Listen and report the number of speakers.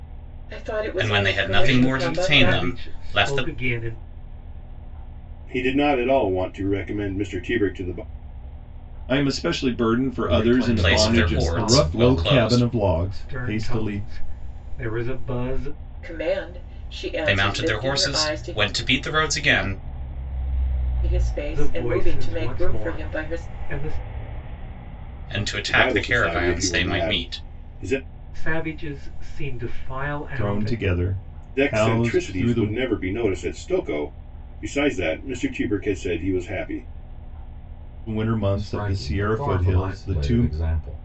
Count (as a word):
six